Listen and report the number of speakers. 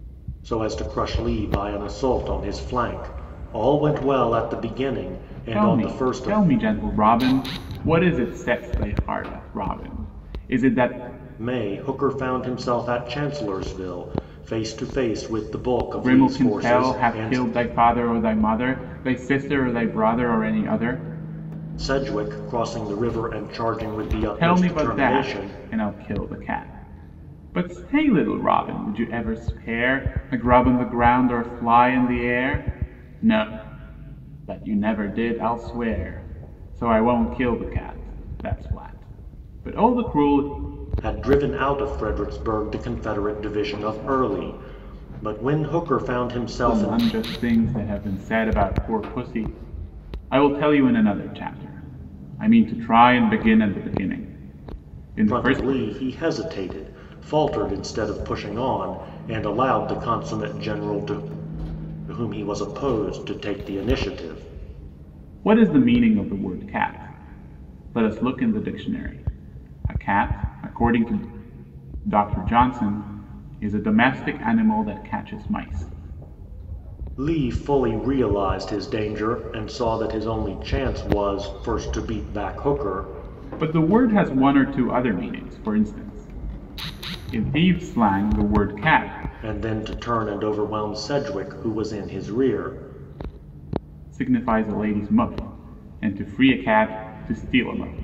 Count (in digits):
2